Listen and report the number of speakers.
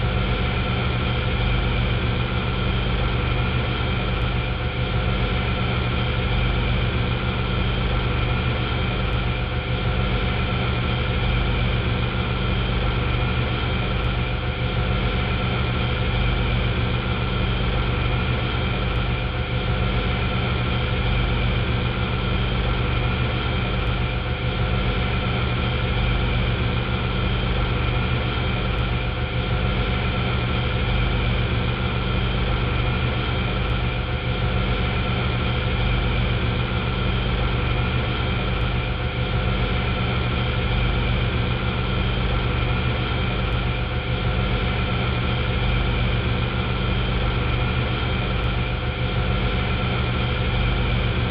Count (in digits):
0